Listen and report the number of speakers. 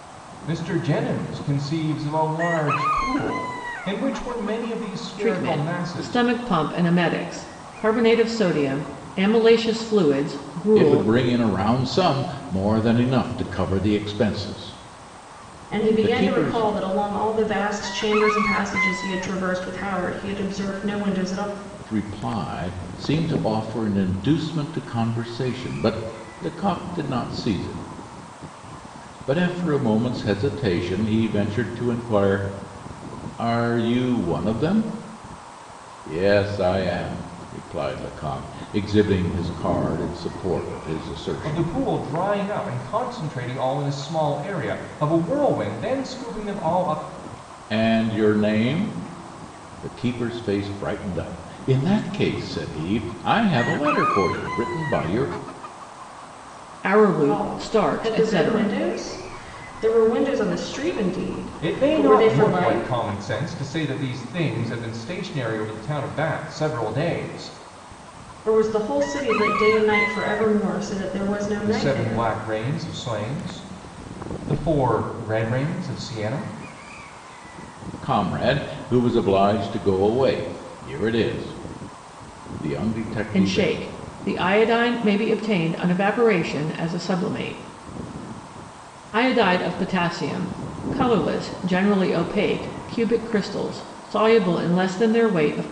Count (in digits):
4